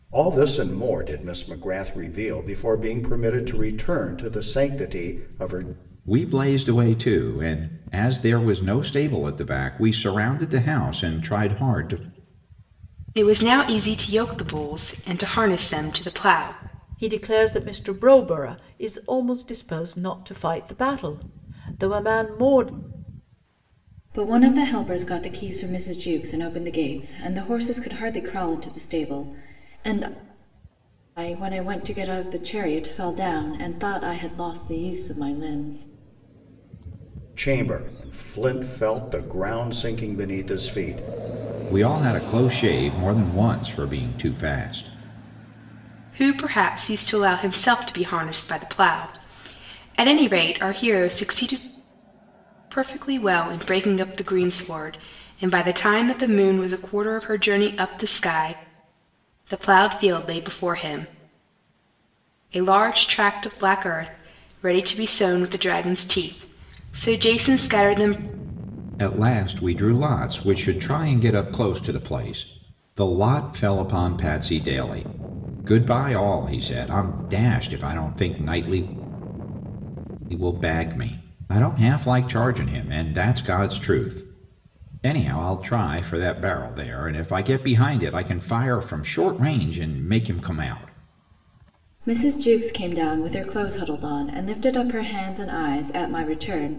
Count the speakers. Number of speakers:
5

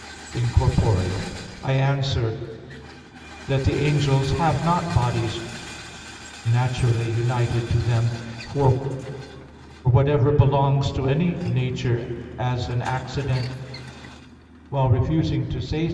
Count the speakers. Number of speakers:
1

